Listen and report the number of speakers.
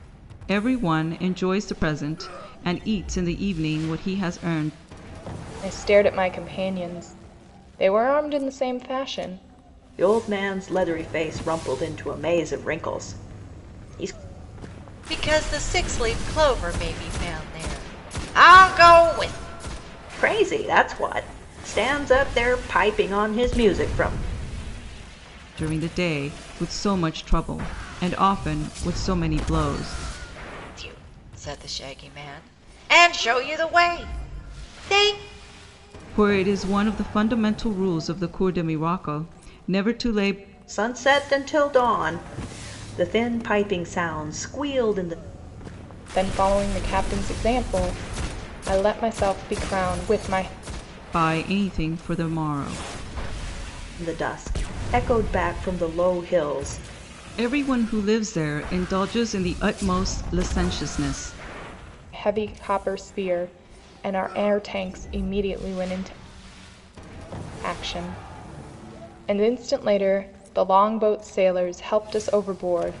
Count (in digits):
4